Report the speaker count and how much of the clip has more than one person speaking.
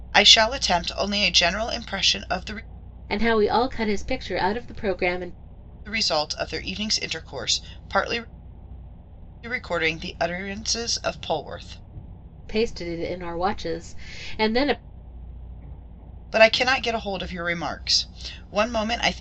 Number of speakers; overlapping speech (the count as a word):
two, no overlap